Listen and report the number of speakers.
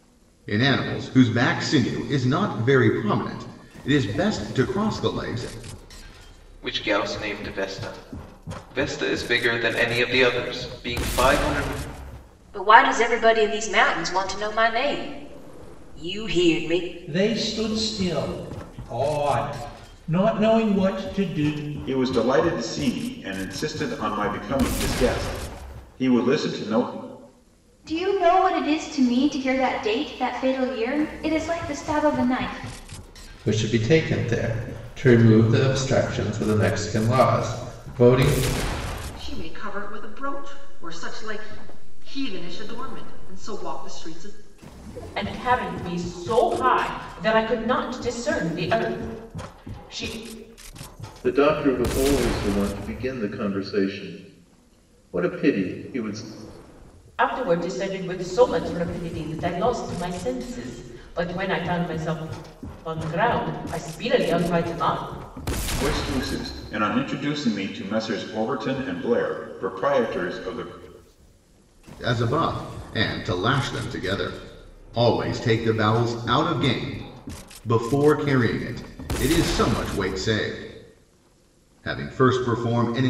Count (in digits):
10